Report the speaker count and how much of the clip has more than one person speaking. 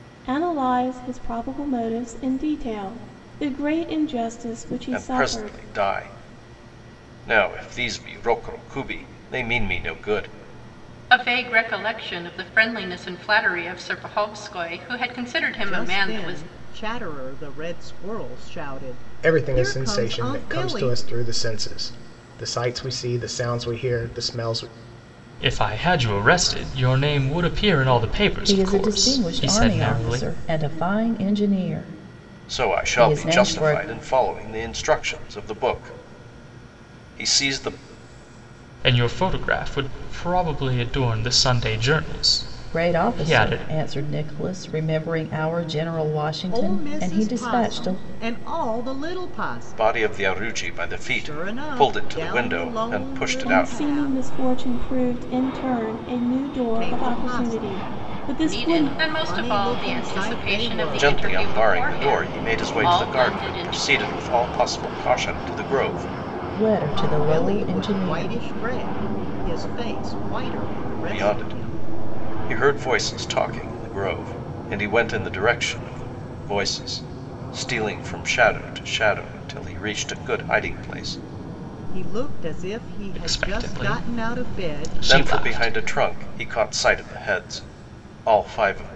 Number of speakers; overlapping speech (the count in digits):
7, about 29%